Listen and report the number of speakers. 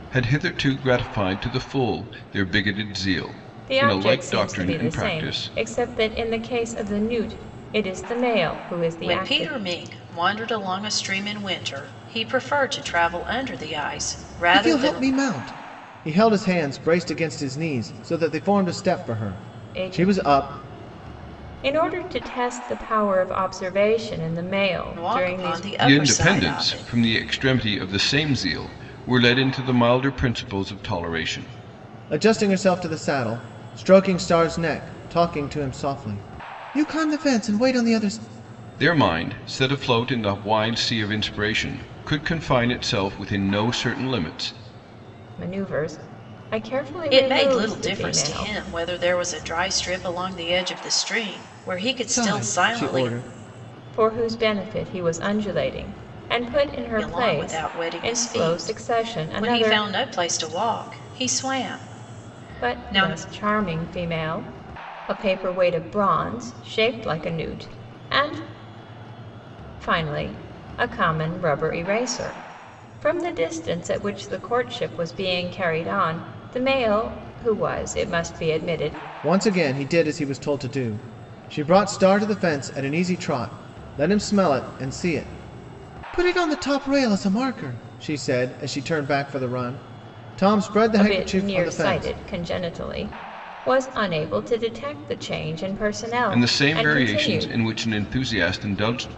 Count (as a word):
four